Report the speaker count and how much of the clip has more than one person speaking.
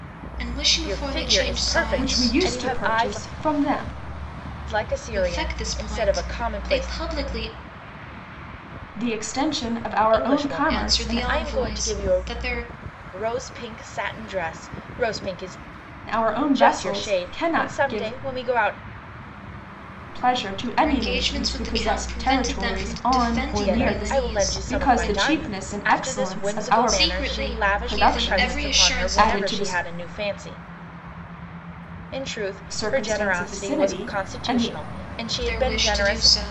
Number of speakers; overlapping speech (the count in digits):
3, about 55%